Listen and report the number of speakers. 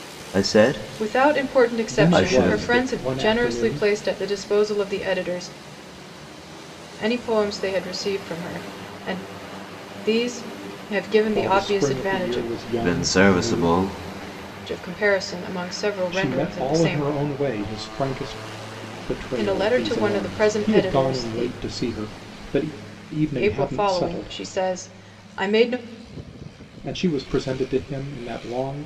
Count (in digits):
3